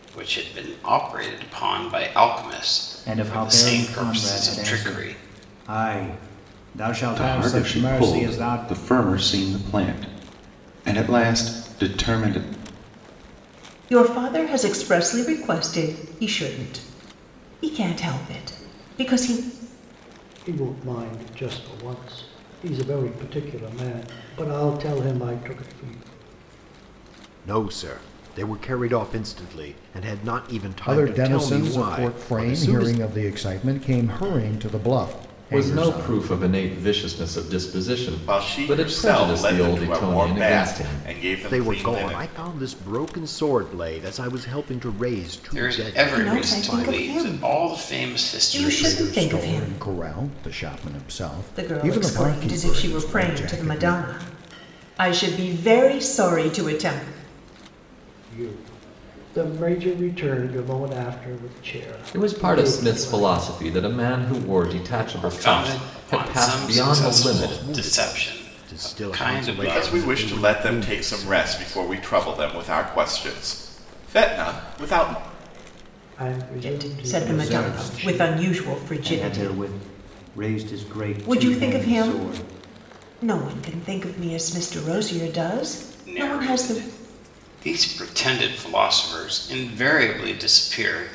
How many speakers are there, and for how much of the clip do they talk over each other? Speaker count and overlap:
nine, about 34%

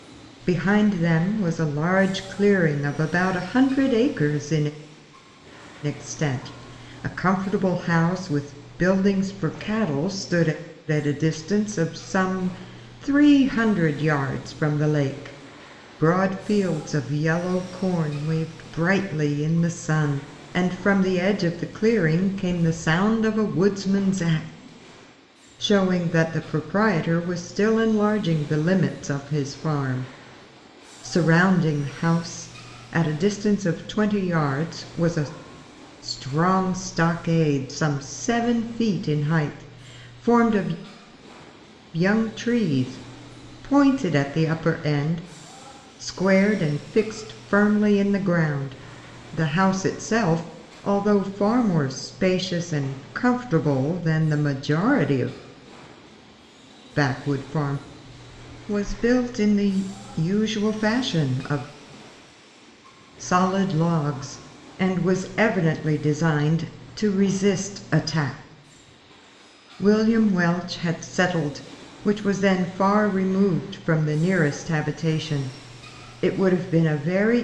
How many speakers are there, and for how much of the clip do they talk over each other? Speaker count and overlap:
one, no overlap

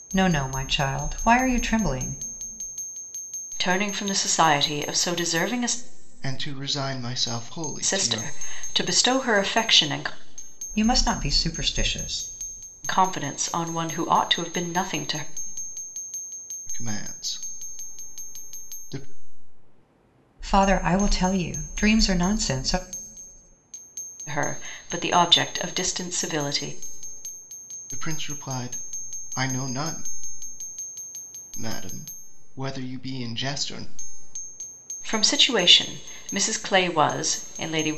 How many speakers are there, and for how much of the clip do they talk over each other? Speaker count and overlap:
three, about 1%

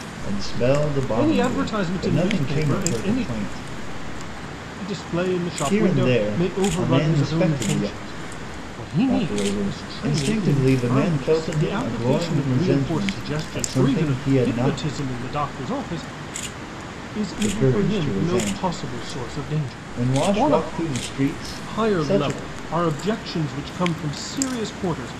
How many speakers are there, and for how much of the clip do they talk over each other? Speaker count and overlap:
two, about 50%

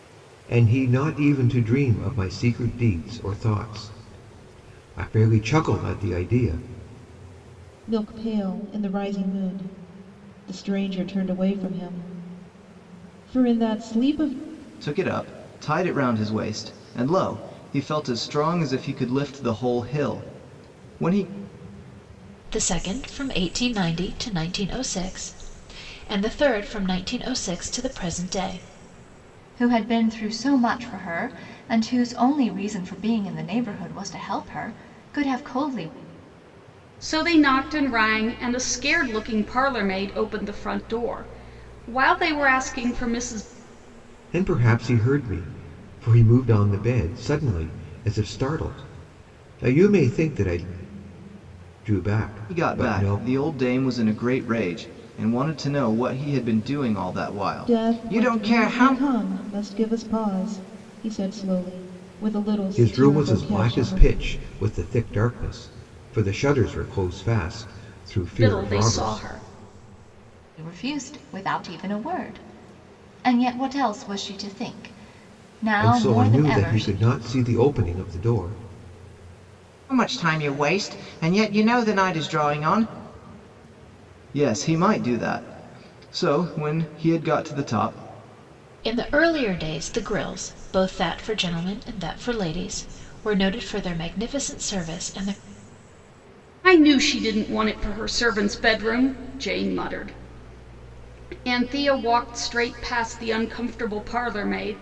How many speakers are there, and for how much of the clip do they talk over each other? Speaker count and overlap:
six, about 5%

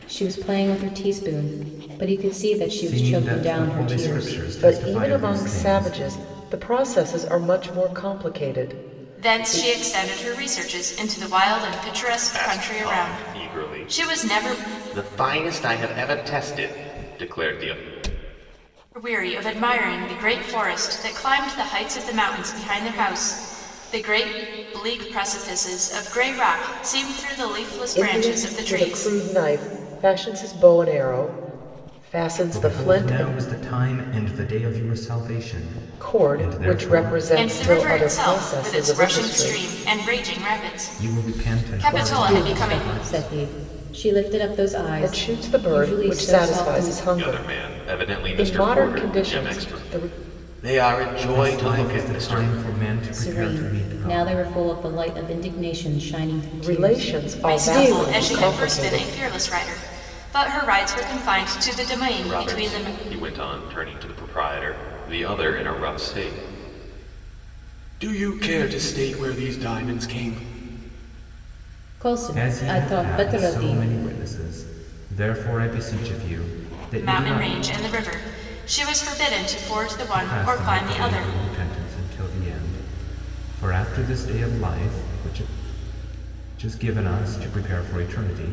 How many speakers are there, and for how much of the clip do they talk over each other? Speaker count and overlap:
five, about 32%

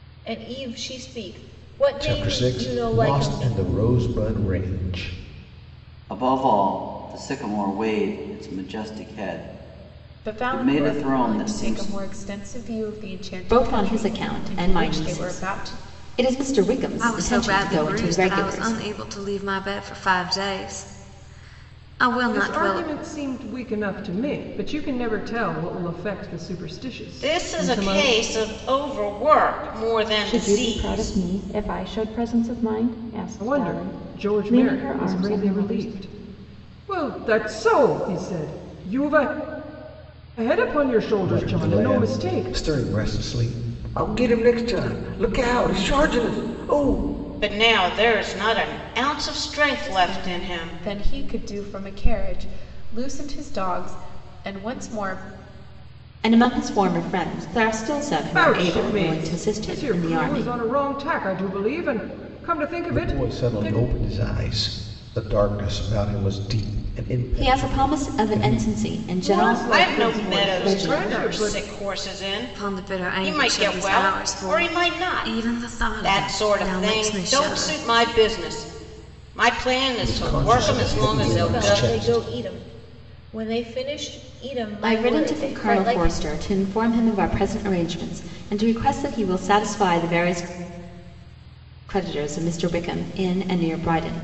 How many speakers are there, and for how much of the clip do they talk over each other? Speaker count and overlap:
nine, about 32%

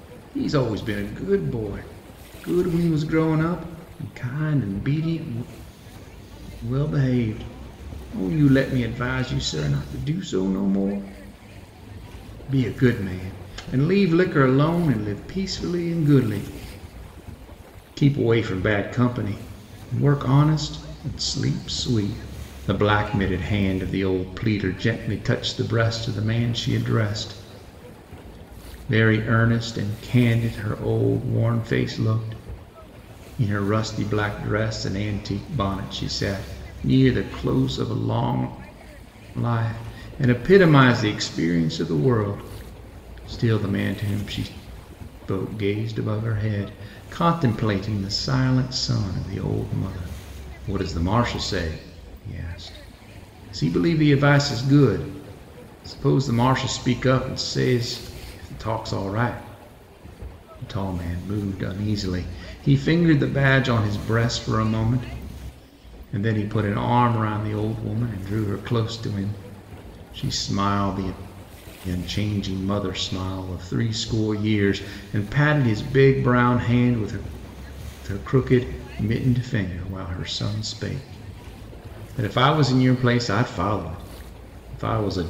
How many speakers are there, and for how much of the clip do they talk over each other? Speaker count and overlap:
one, no overlap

